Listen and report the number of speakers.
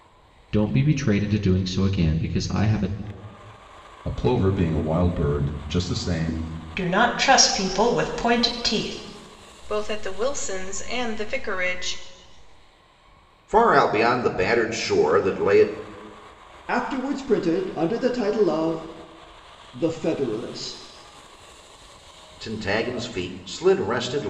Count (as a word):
six